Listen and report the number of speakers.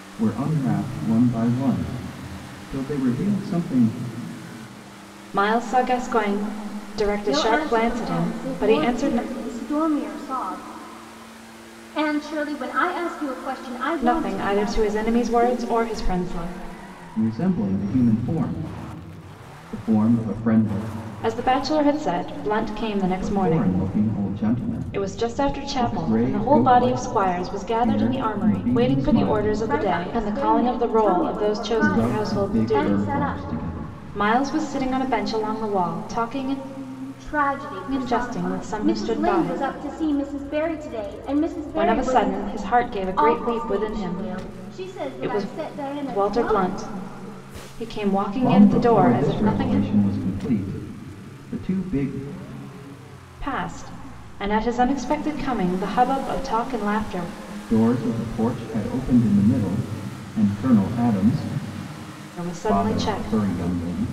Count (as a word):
three